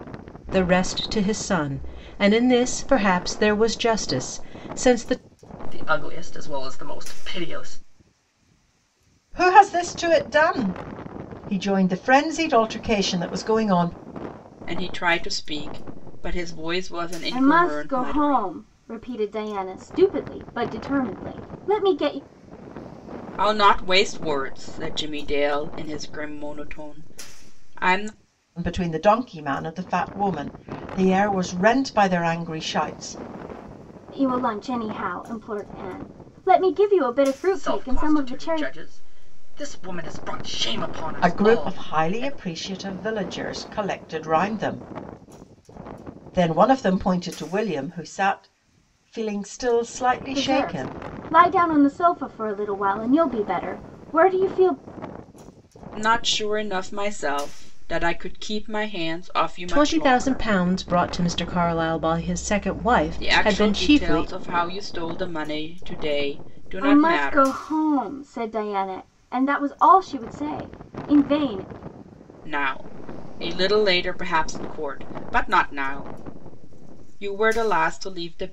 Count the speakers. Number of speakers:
5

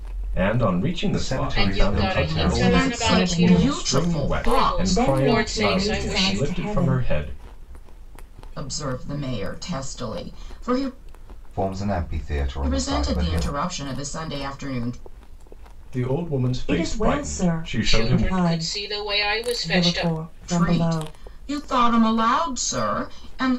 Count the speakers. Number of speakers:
5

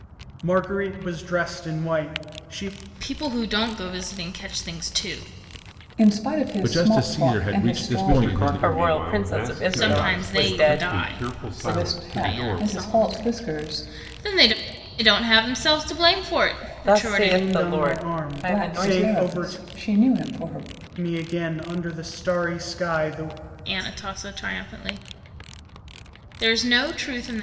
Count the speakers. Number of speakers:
6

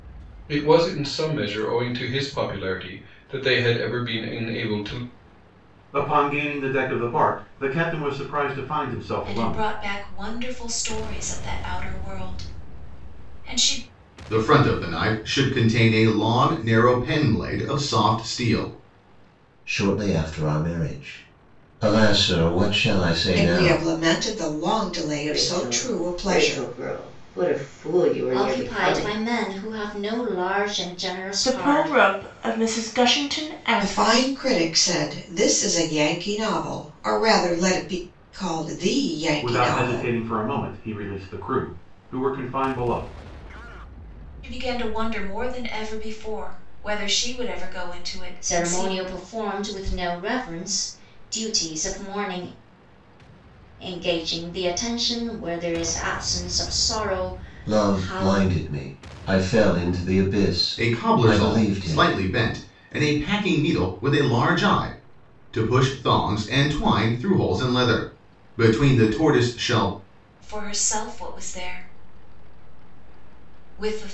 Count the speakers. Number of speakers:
9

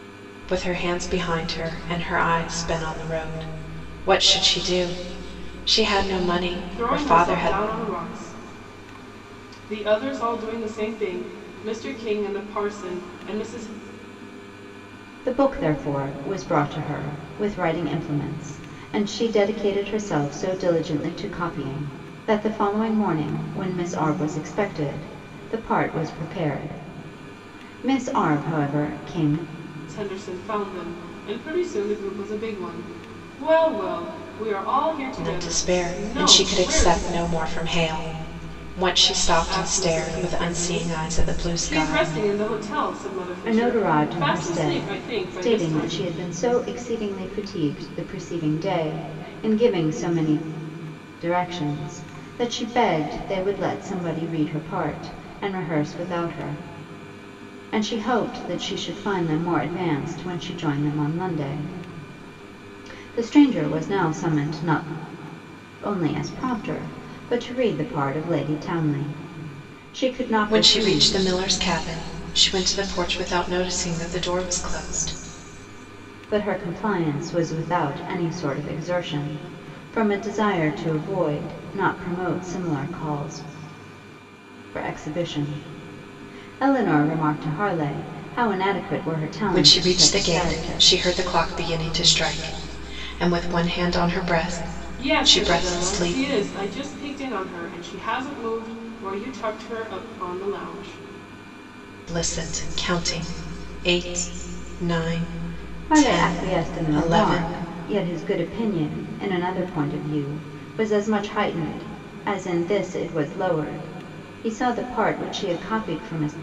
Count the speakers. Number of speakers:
3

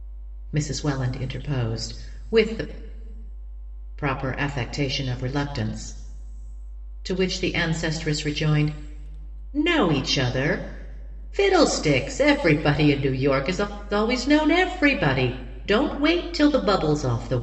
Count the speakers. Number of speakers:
1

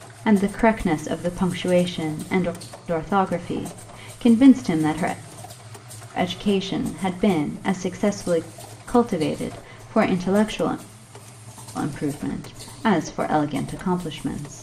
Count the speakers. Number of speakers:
1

